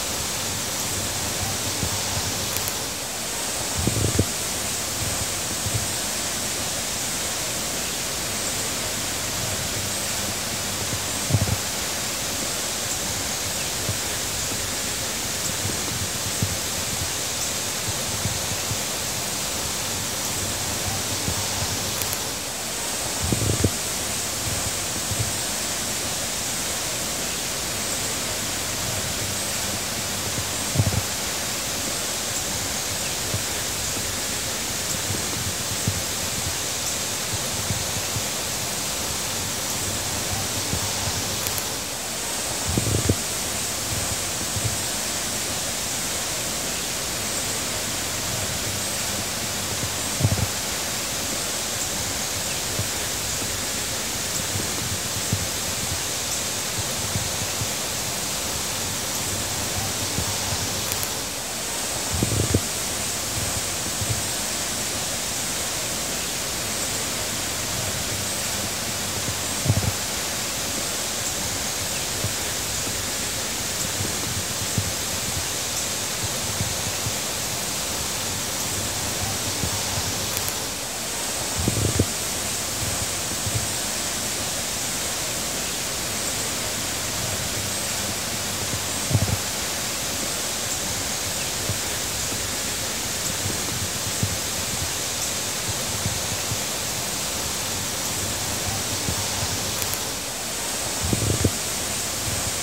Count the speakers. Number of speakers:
zero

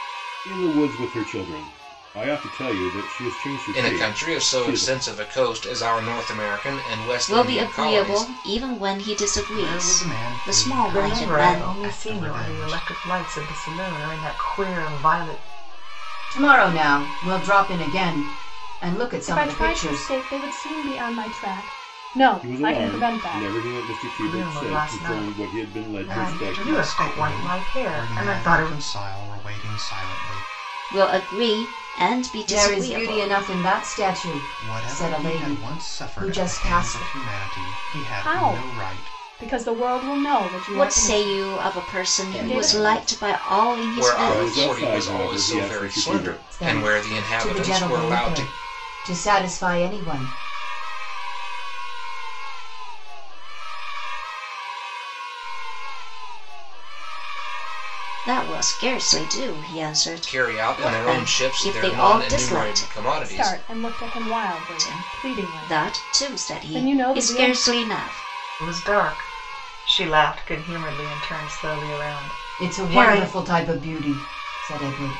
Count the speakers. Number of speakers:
eight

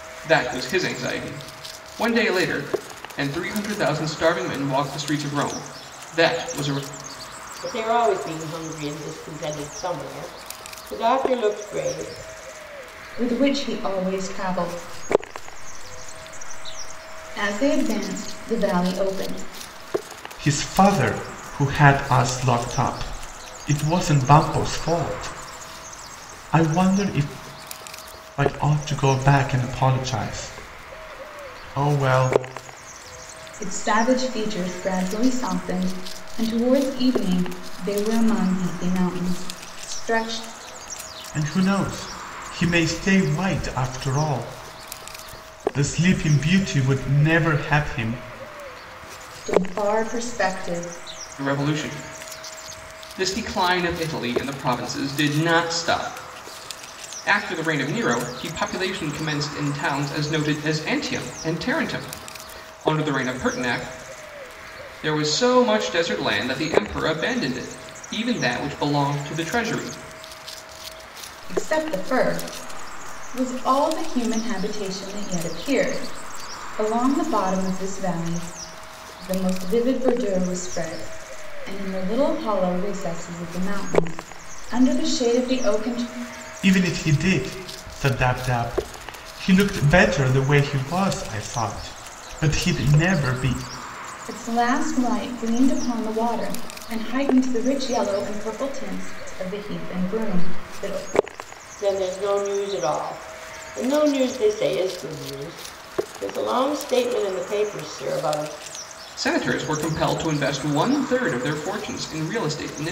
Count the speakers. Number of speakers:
four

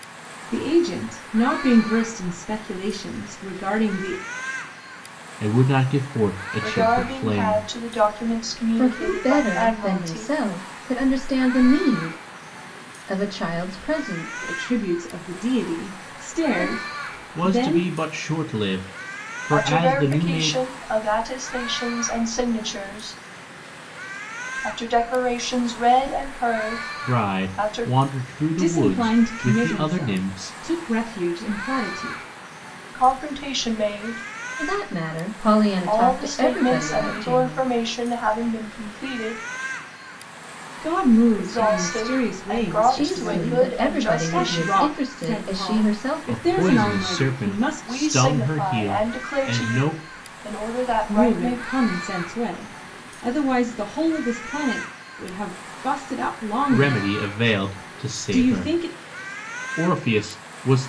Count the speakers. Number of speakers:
four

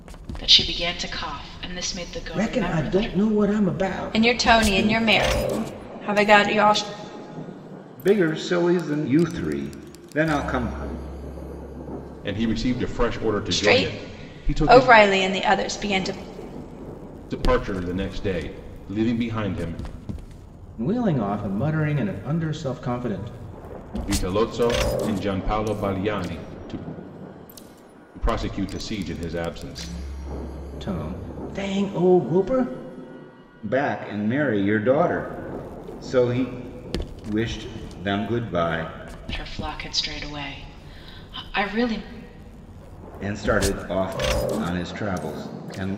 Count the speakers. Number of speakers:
five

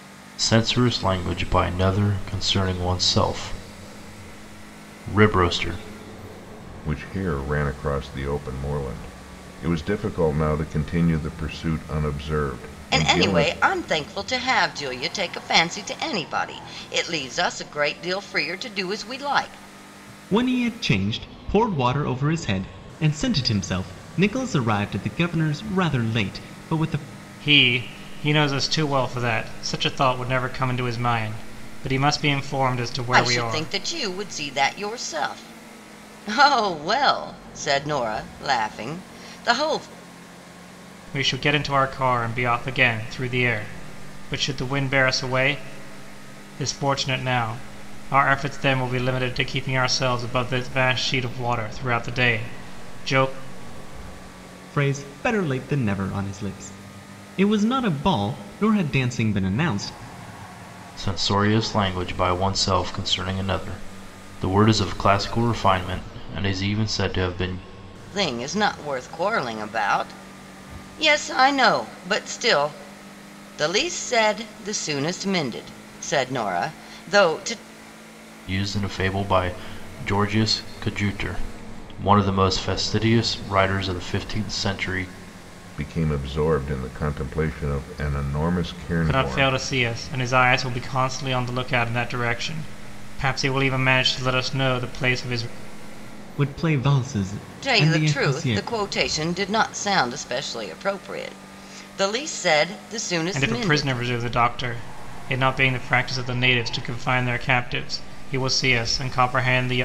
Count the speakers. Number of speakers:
five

